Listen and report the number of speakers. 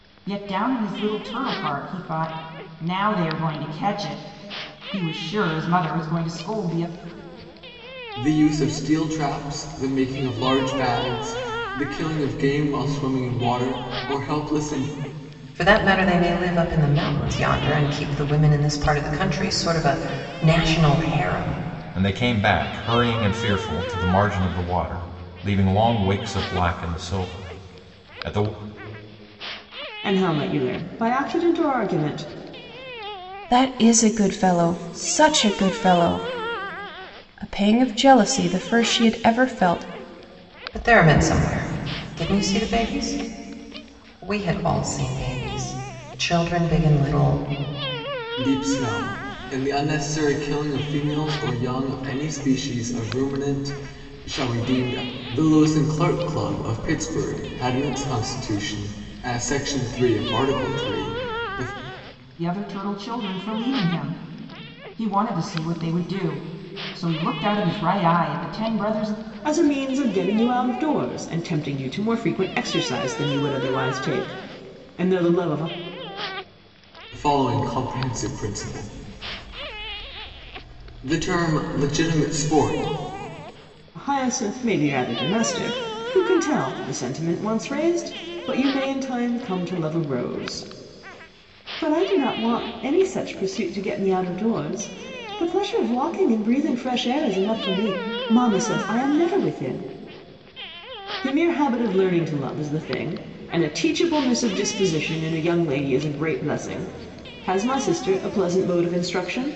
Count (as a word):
six